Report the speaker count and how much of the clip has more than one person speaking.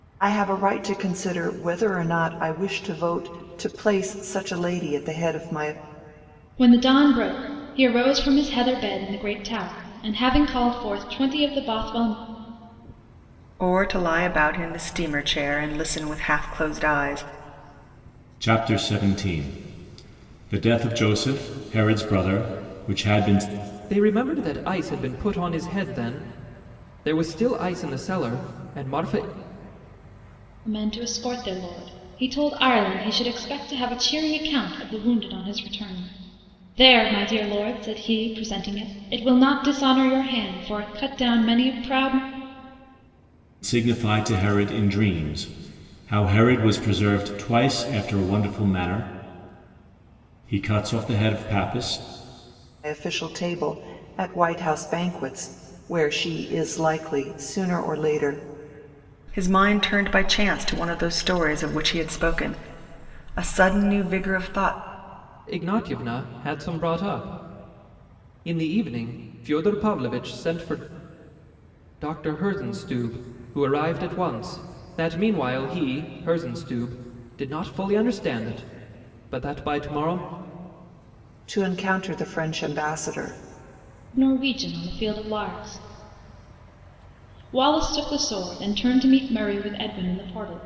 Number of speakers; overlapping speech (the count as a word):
five, no overlap